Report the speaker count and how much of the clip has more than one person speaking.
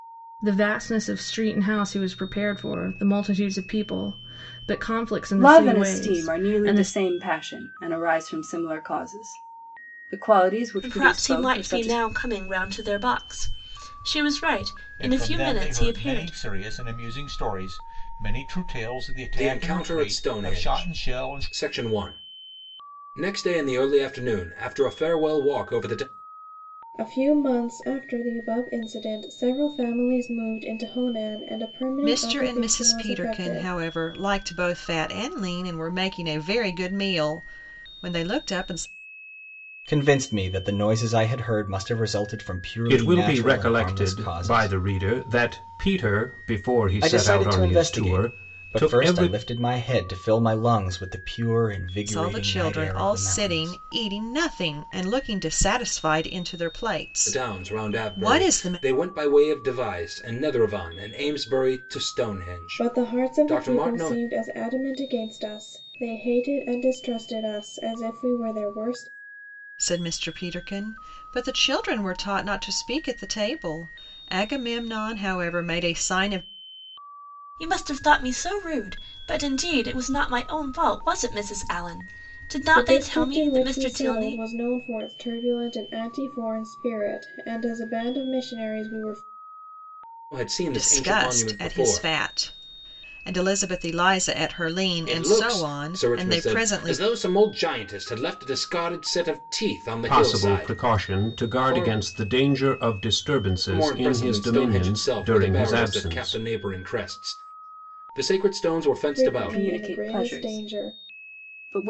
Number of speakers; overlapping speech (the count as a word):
nine, about 26%